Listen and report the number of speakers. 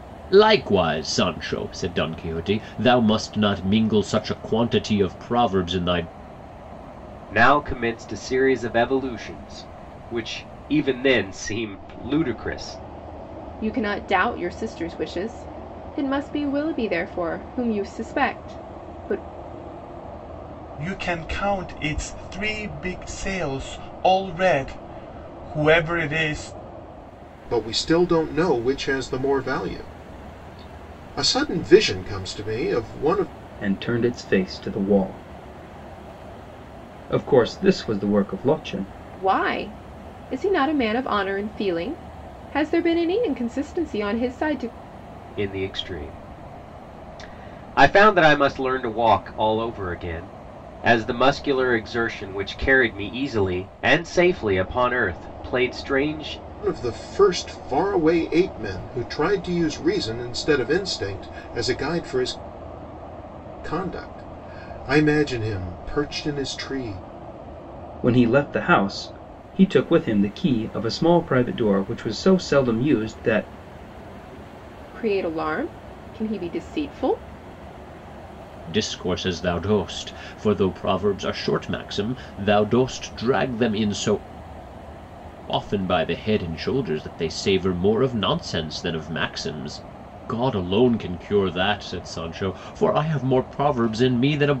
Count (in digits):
6